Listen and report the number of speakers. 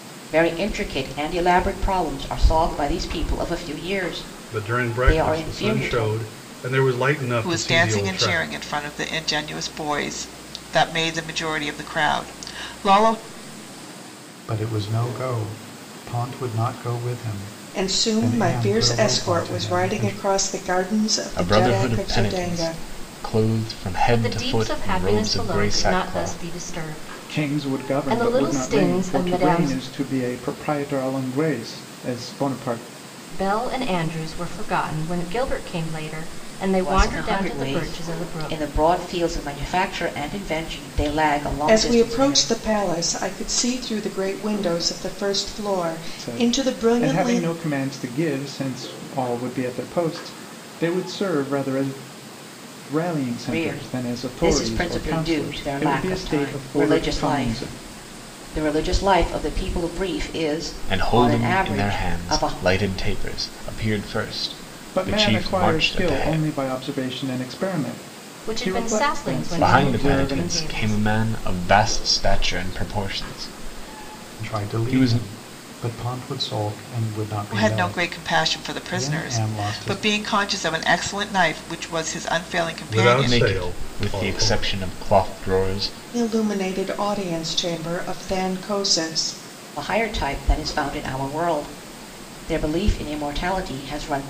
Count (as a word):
eight